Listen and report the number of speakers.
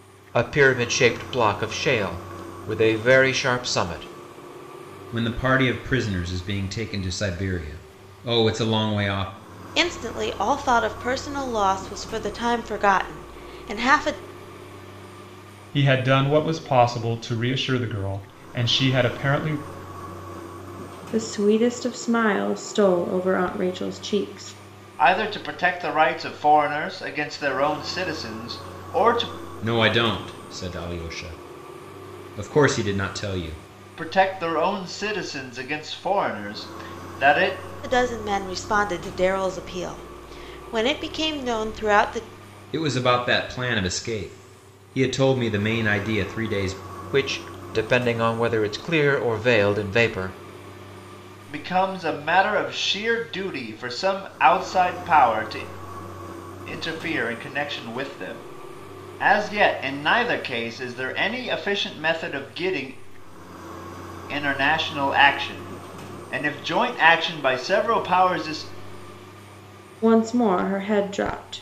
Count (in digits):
6